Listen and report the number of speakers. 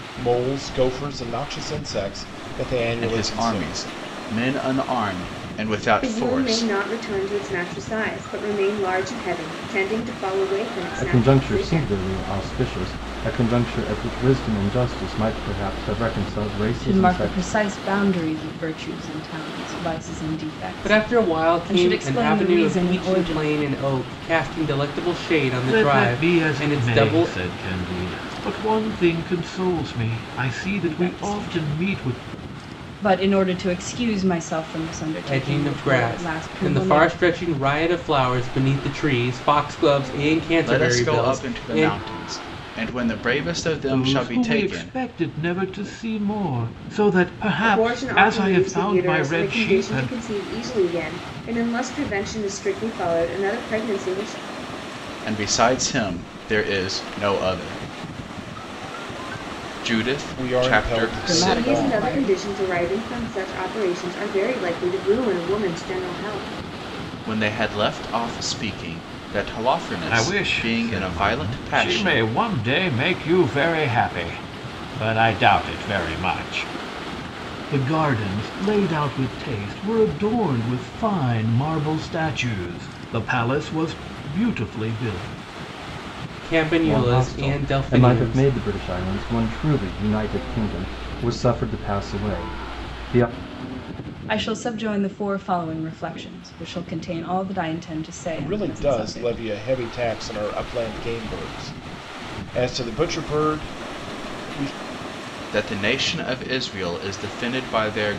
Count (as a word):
seven